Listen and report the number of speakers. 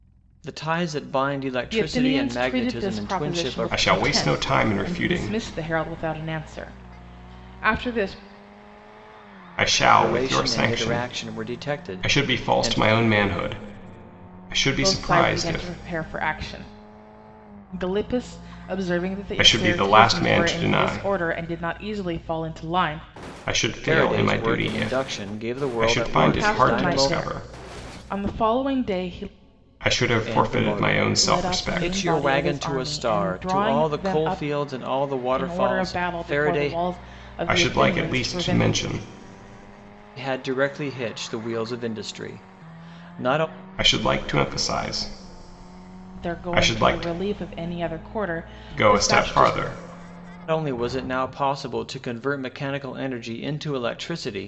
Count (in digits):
3